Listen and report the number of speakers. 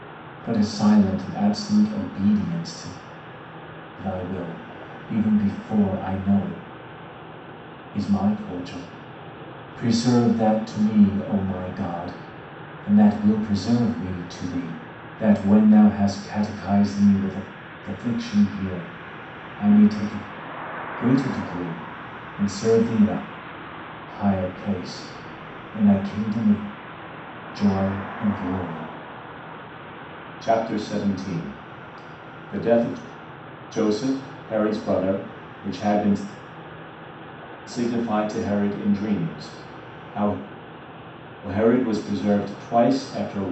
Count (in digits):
1